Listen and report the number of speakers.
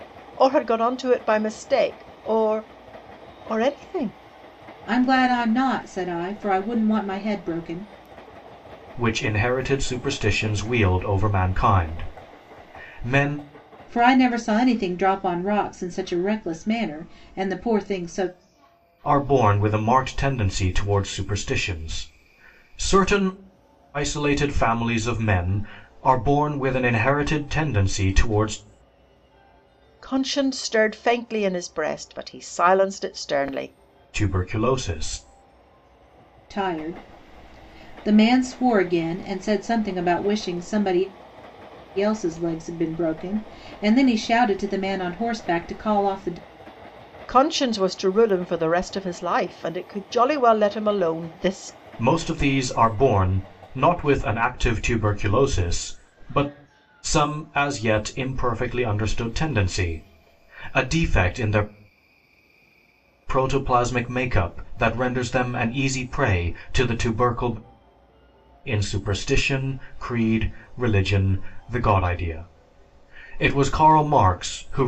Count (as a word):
three